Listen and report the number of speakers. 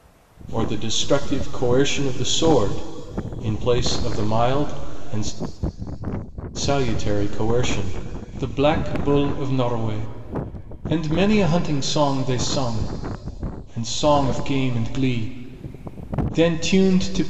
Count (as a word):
one